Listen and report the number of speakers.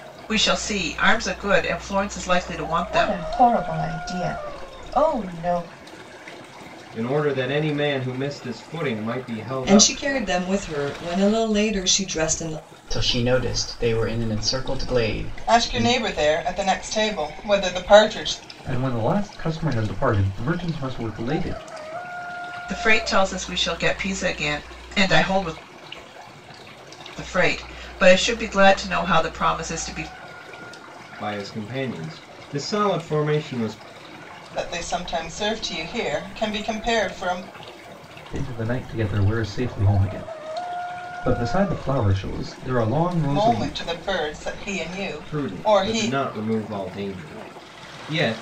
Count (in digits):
7